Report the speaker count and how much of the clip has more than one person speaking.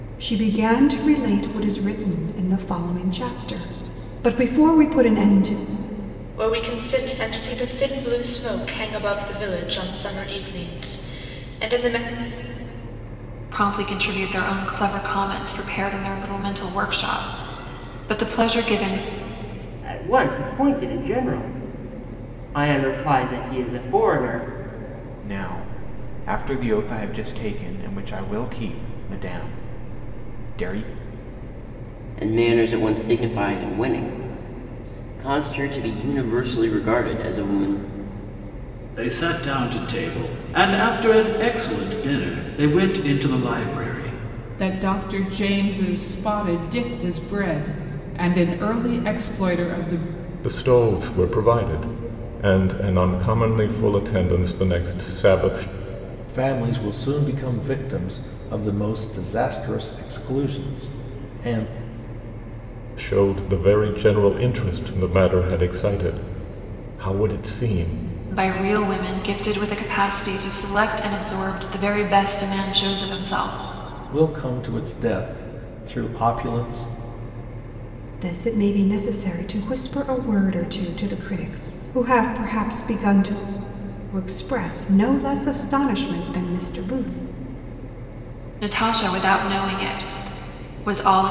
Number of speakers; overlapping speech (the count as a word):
ten, no overlap